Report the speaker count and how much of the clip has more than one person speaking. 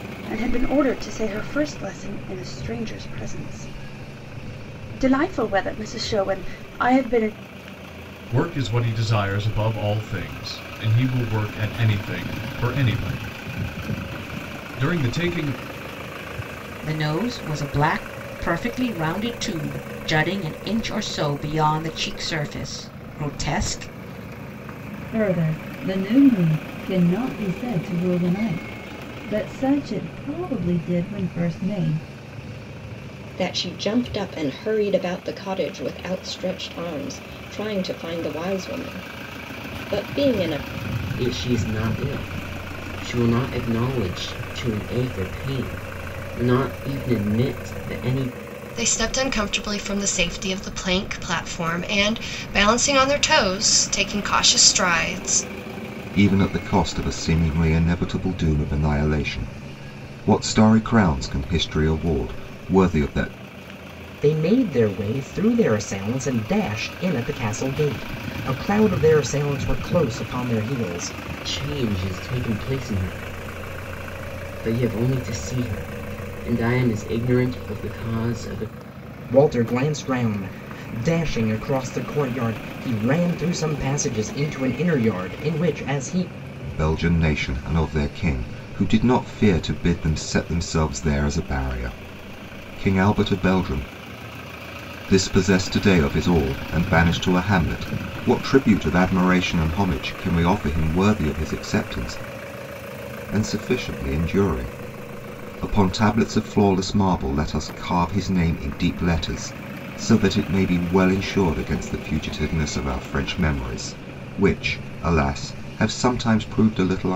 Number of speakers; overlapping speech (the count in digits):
9, no overlap